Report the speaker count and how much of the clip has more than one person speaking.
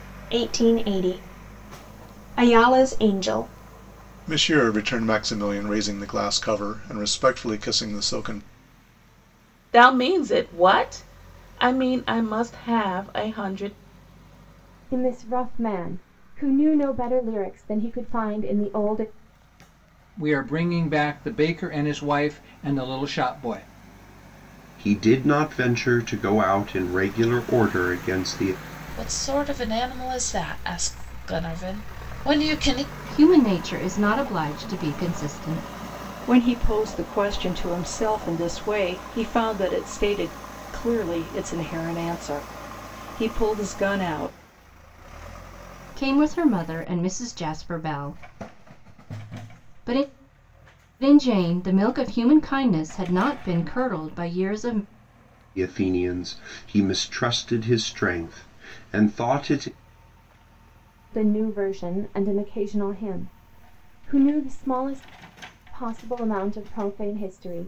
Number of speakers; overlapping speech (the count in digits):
9, no overlap